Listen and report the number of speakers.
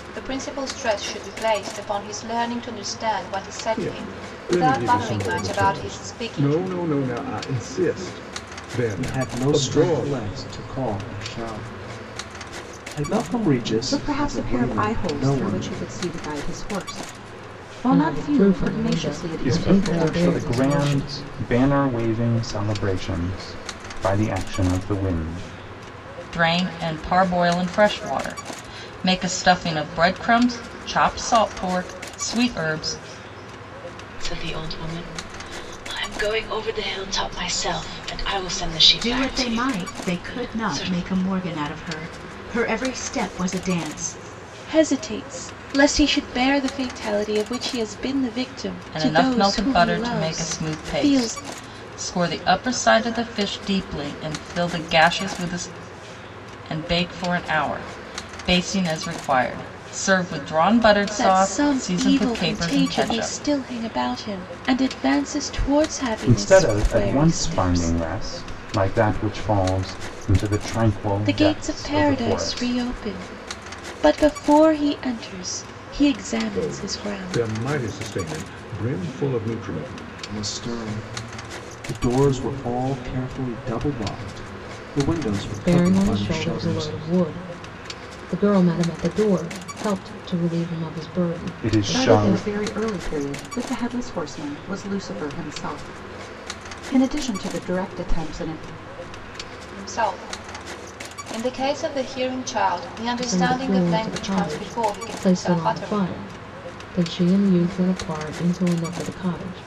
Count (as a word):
ten